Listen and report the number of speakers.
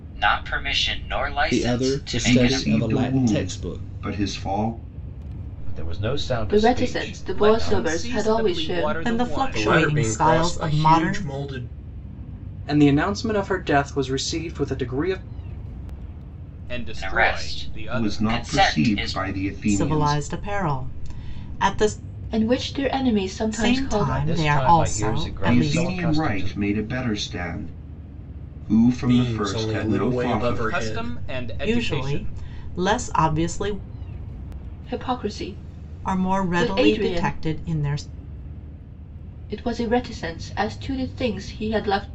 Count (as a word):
nine